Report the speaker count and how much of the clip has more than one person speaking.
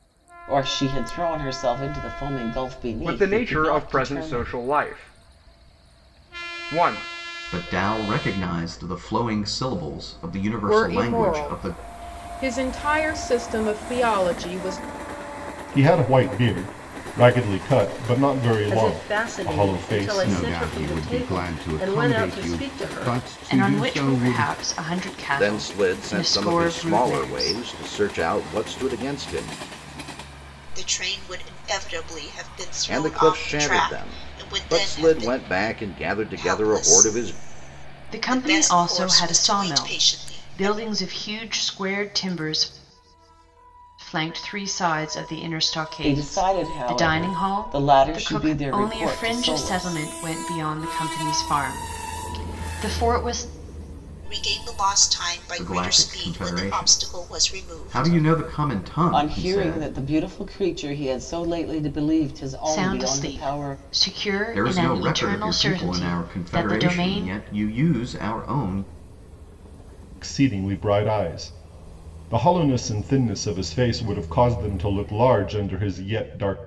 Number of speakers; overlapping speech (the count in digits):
10, about 37%